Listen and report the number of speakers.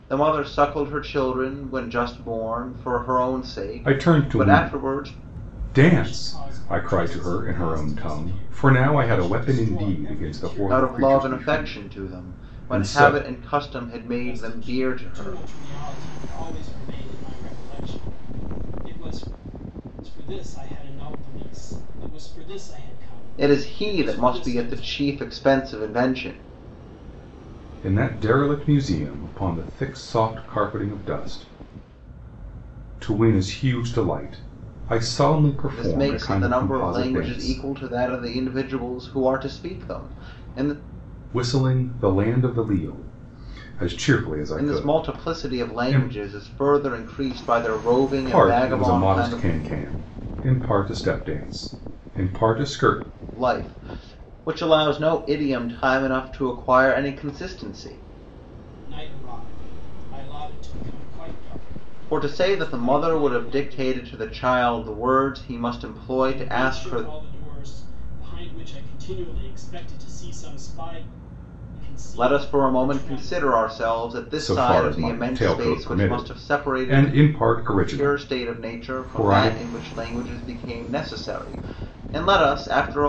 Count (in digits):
3